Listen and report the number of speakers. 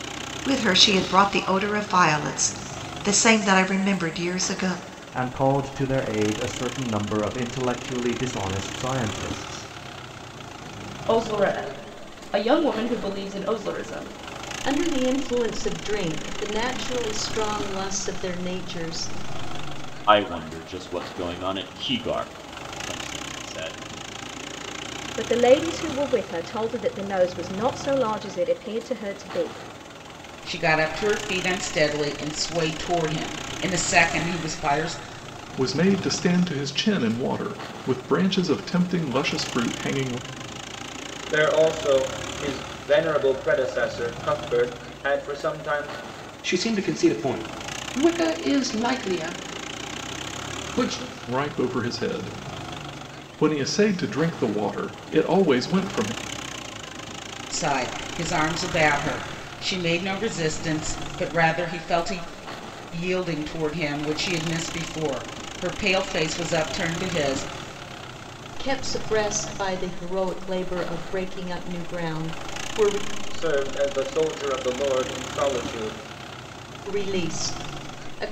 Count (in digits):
10